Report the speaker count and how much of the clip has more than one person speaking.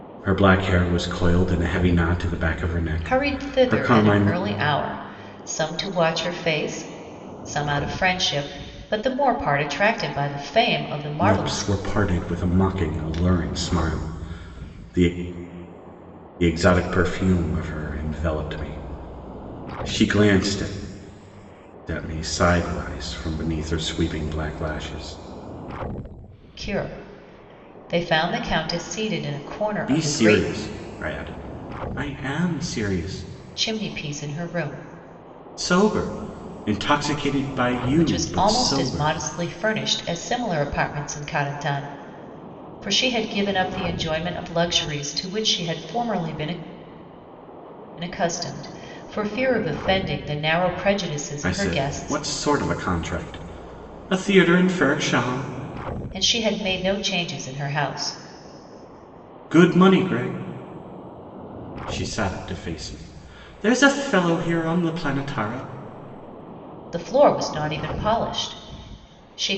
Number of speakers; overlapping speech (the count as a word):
two, about 7%